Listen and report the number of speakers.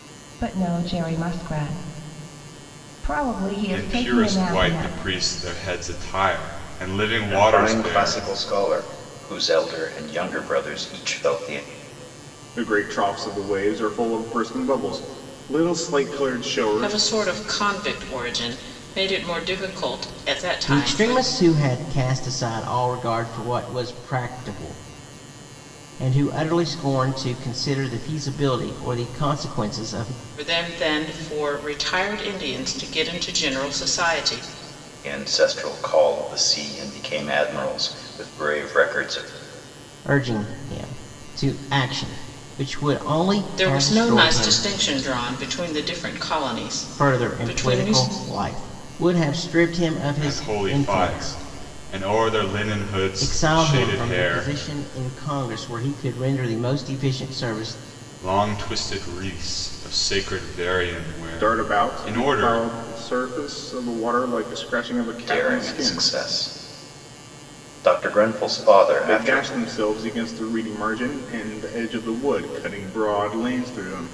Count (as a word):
six